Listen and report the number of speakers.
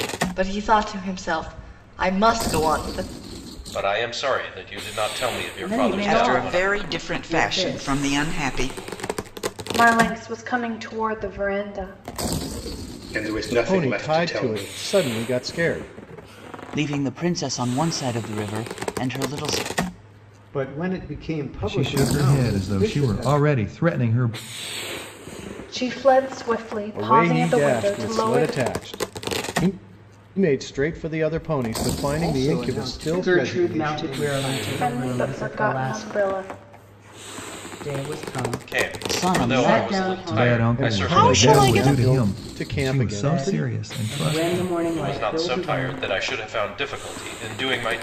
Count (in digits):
10